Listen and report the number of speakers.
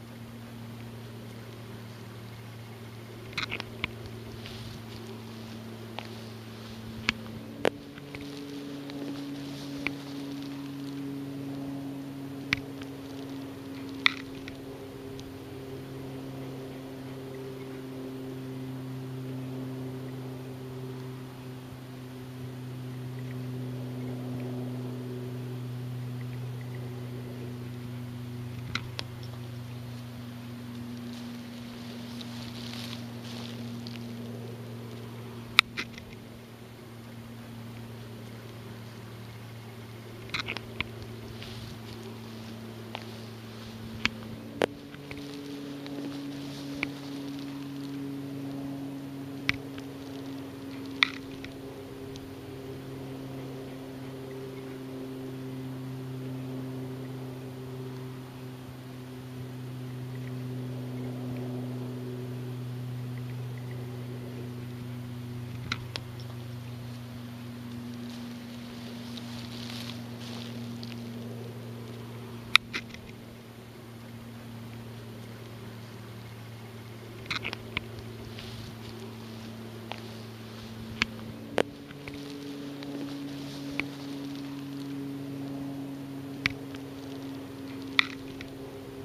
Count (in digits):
0